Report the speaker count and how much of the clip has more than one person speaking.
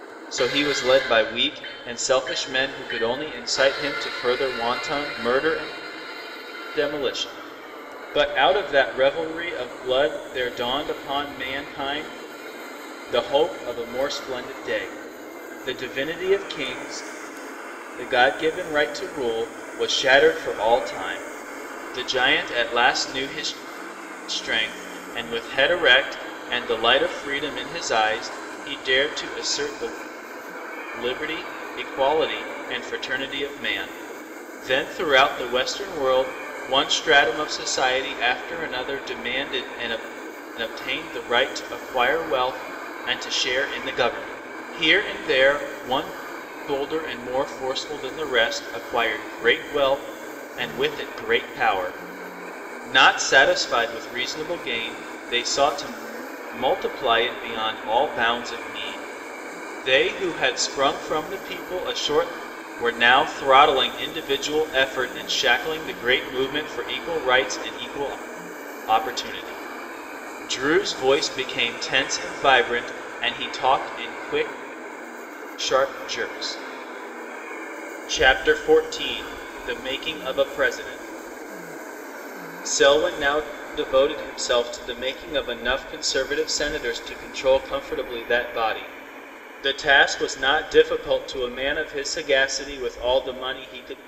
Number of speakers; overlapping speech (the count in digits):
1, no overlap